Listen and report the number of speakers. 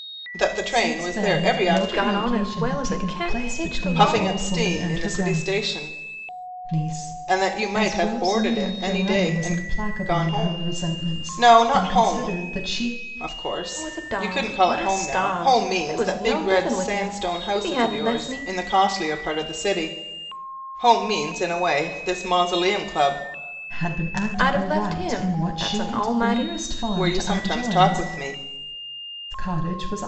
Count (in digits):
3